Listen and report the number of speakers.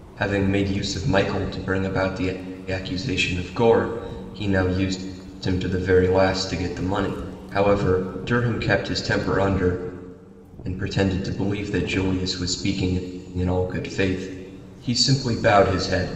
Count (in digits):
1